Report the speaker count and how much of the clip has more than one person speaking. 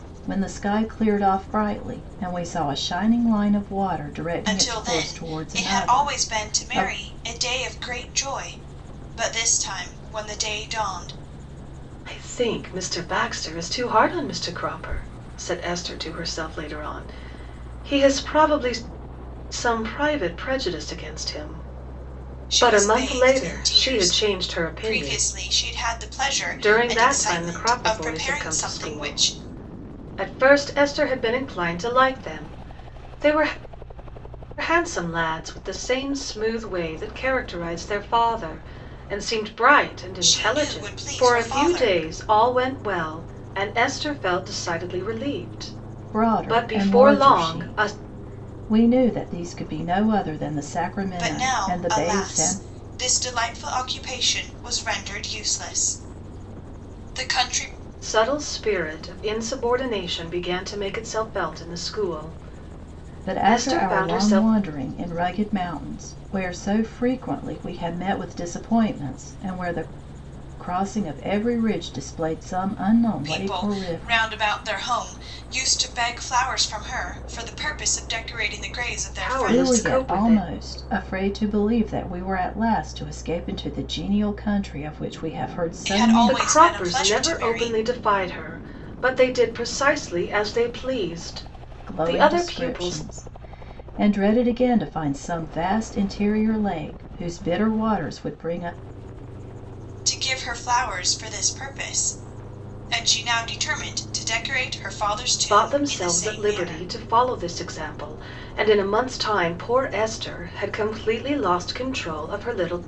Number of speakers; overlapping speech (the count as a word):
three, about 19%